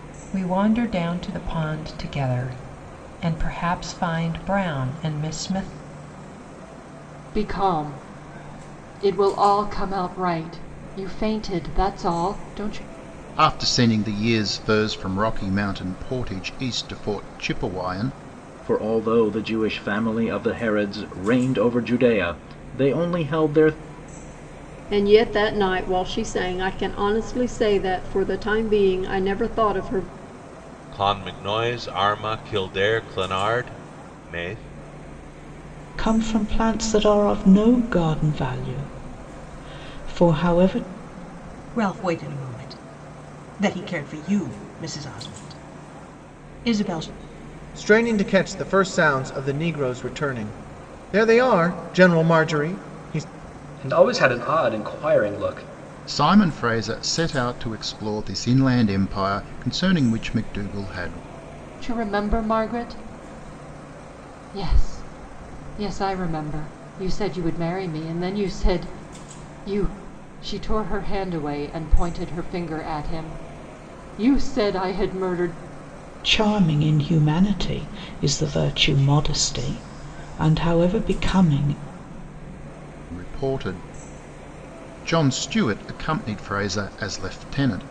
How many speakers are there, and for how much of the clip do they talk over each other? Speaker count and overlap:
ten, no overlap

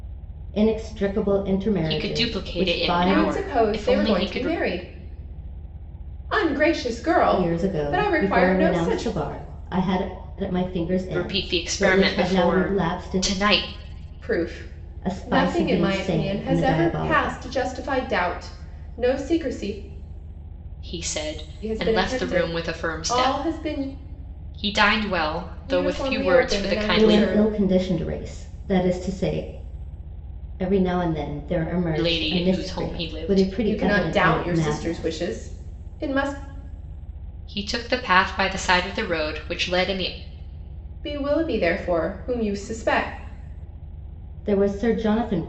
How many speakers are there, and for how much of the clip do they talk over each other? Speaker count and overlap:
three, about 35%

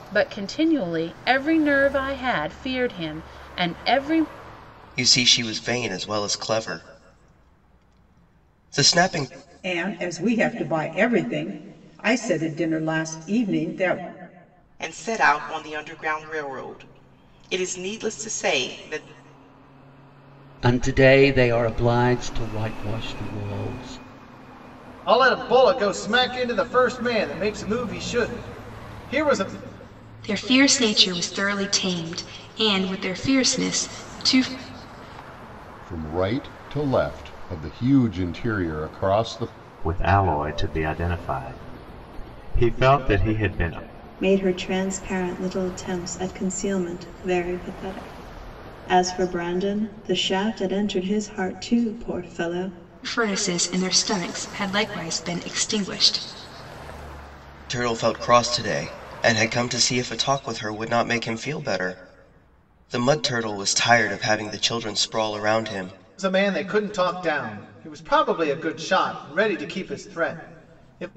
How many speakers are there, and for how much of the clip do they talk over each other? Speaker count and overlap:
ten, no overlap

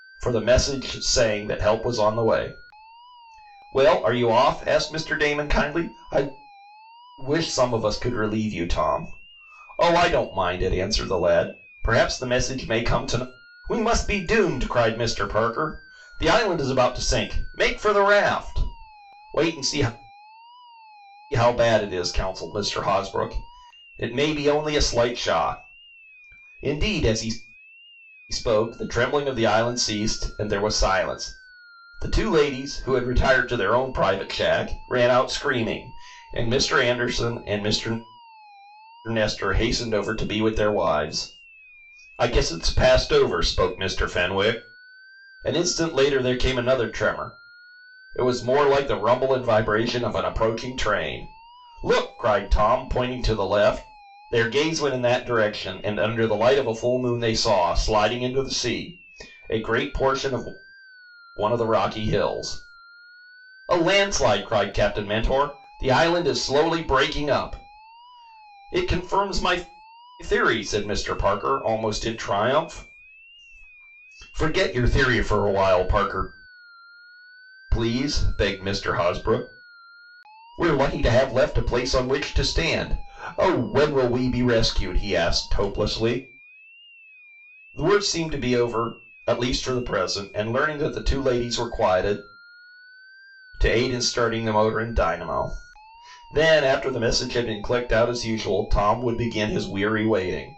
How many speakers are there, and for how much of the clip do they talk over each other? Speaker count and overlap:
one, no overlap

